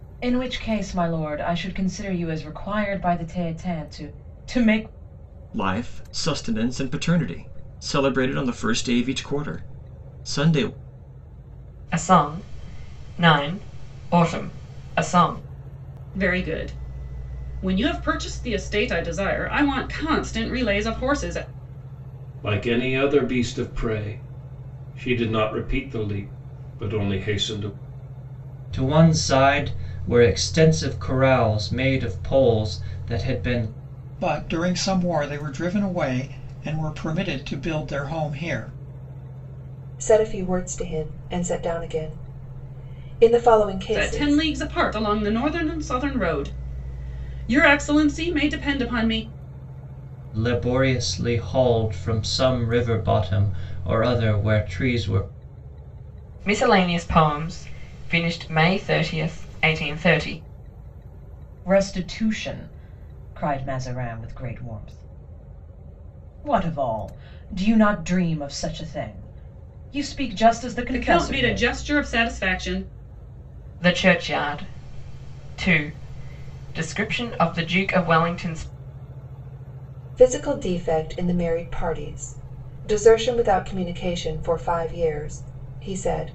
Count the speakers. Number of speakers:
8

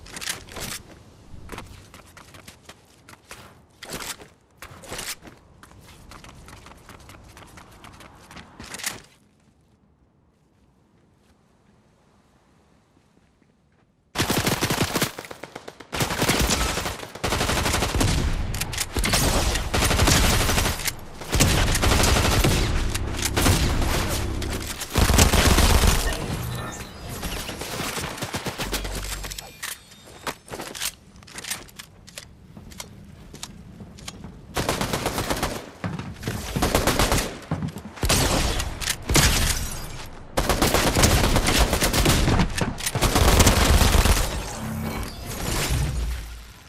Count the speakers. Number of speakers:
0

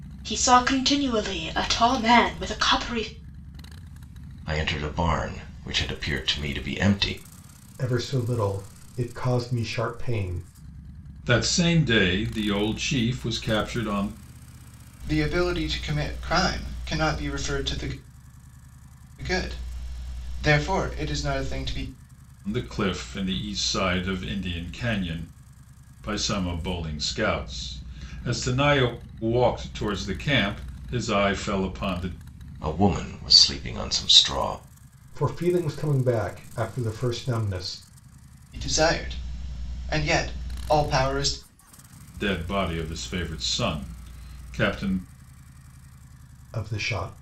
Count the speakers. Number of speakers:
5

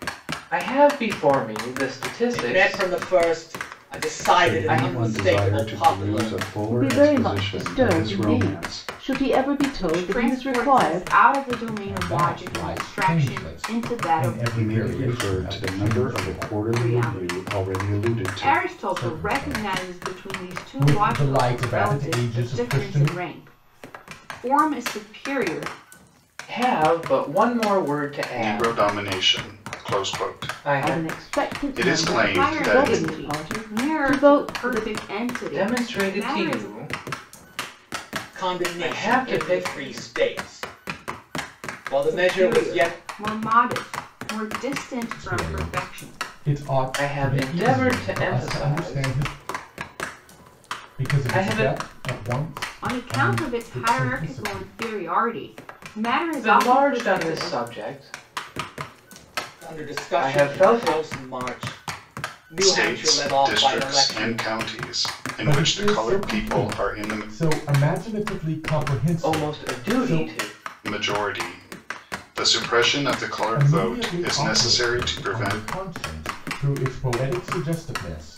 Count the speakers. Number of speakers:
6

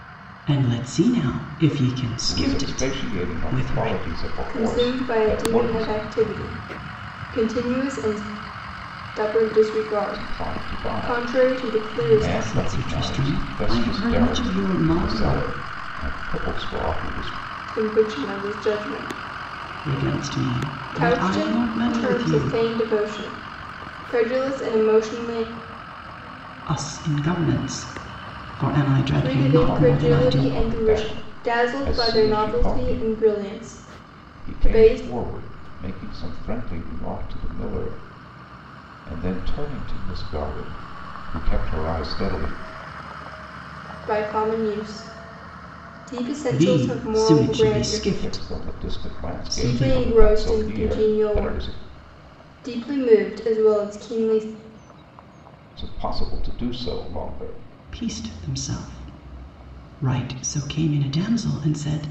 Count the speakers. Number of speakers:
3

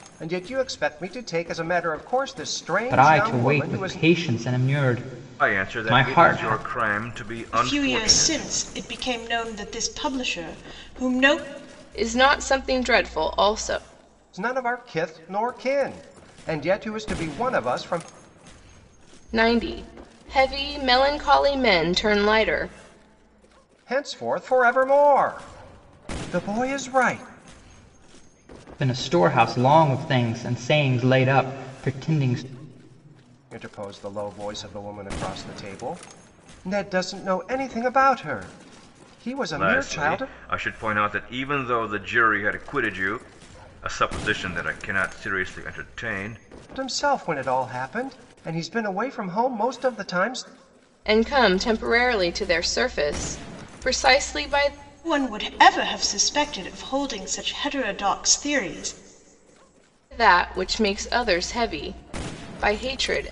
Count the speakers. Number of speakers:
5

